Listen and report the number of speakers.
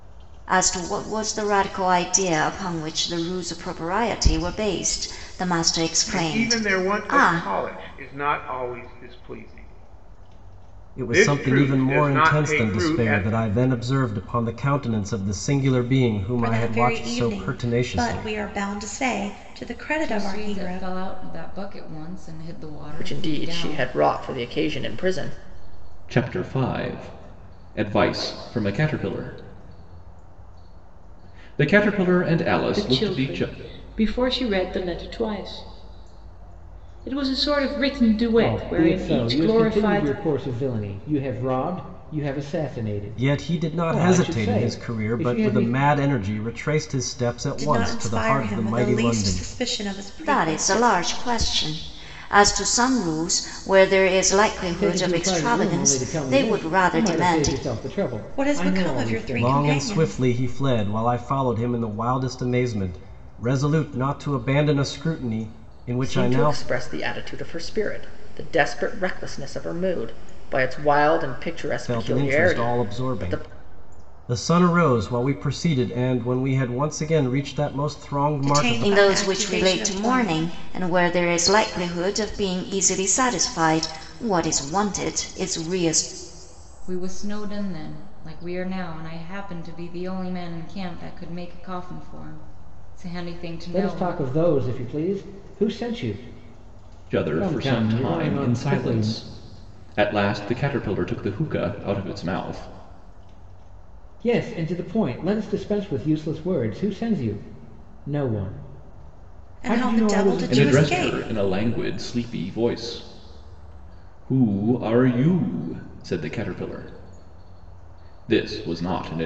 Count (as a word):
nine